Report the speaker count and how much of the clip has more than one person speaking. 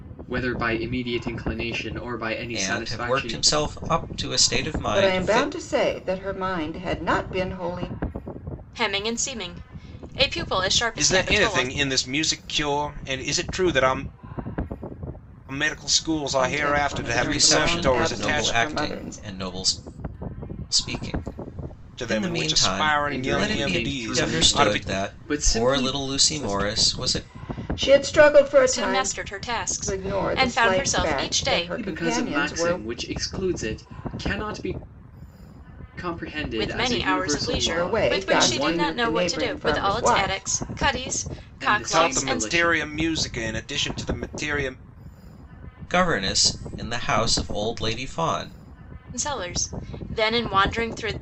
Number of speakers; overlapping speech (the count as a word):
five, about 37%